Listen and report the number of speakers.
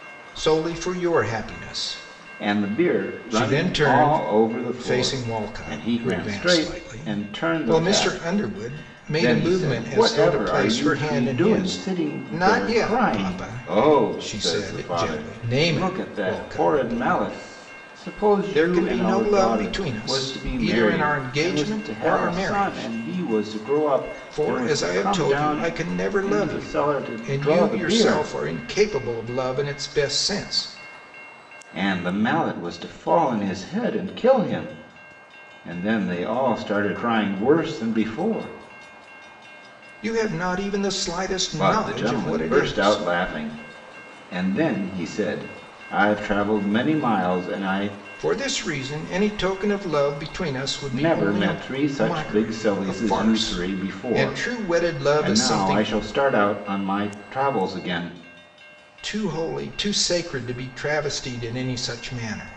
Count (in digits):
2